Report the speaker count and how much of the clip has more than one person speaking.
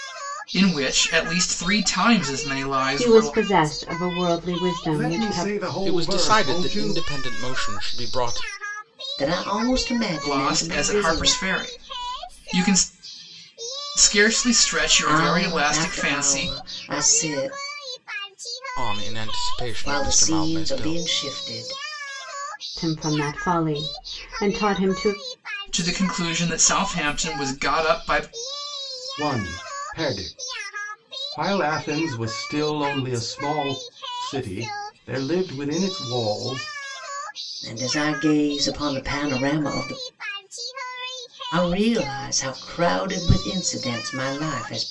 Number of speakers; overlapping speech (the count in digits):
5, about 14%